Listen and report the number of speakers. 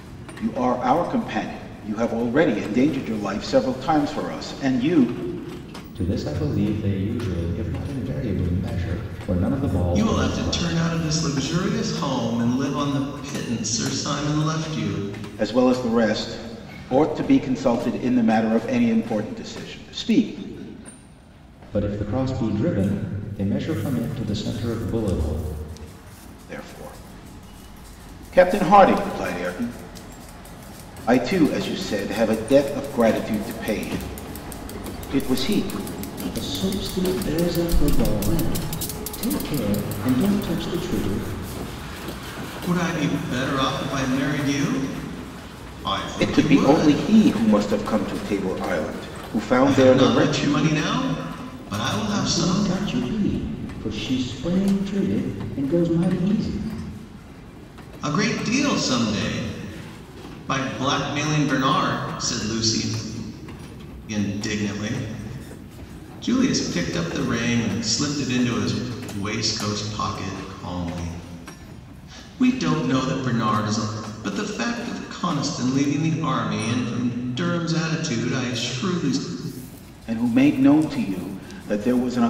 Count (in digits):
3